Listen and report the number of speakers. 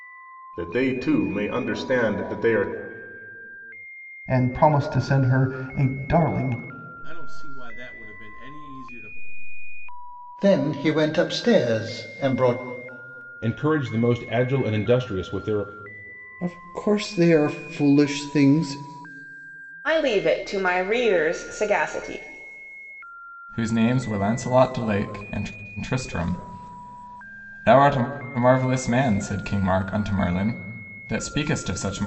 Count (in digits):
8